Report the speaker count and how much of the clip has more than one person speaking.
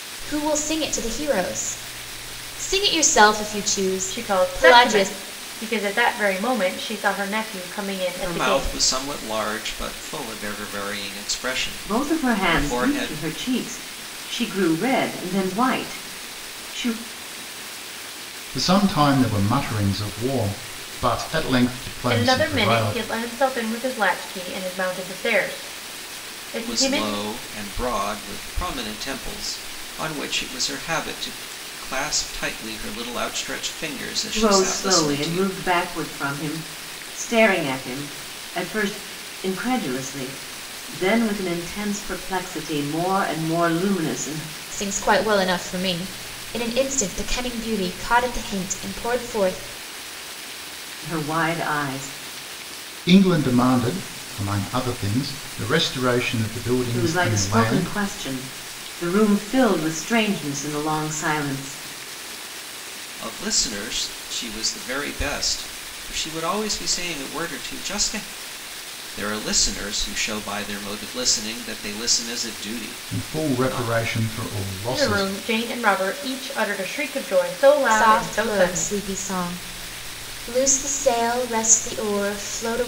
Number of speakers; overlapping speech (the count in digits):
5, about 11%